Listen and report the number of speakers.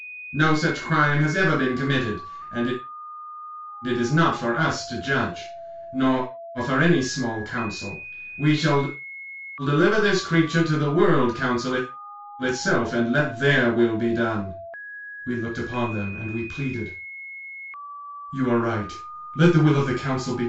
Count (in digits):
1